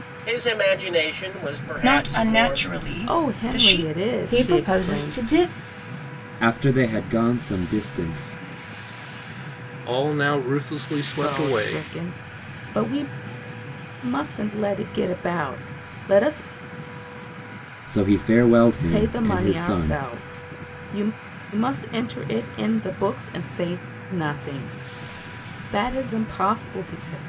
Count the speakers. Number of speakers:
six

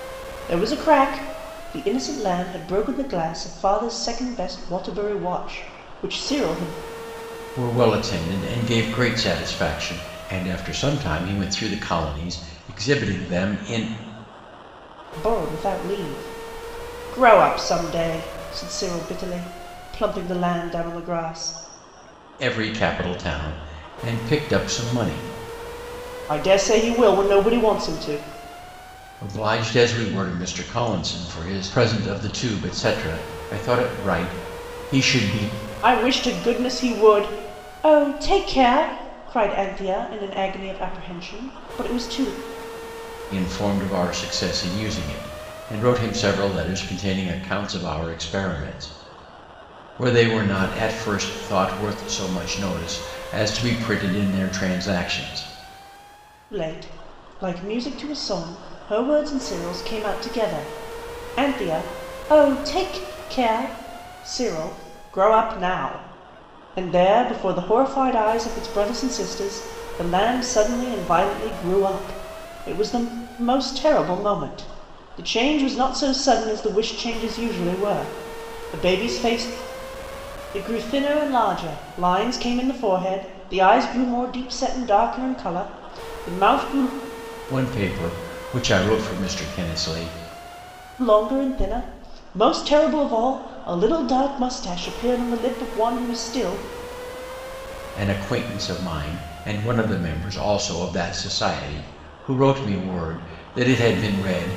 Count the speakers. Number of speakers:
two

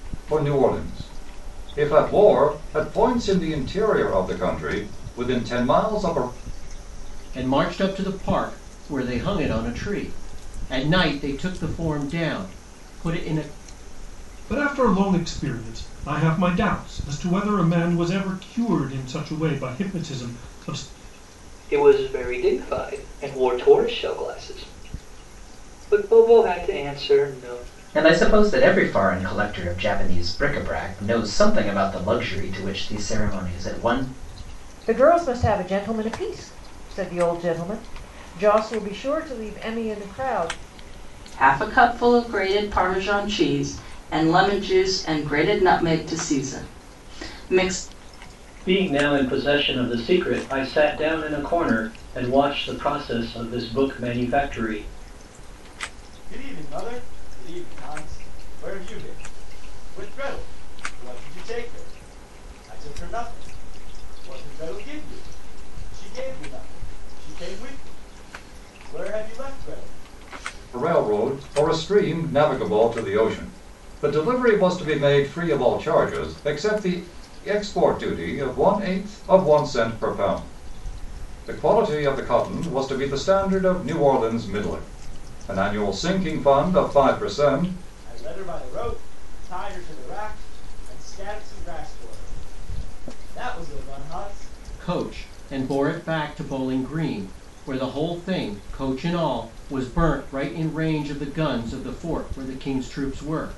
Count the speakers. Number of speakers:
nine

